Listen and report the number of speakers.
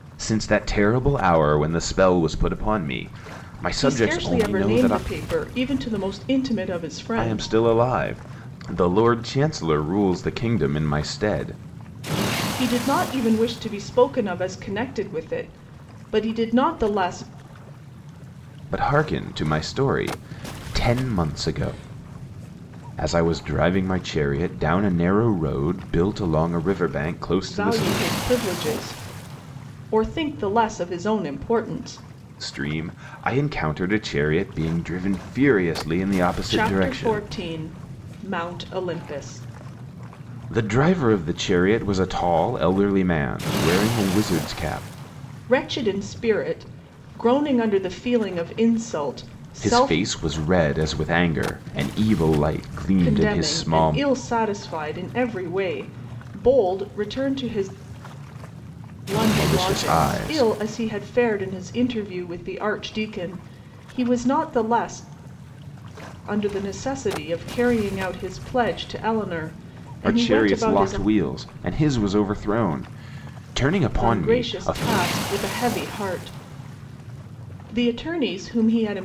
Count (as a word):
two